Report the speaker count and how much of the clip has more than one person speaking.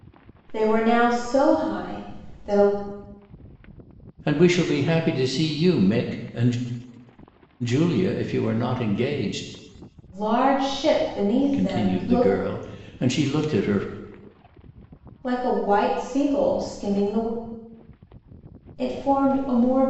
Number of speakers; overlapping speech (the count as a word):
two, about 5%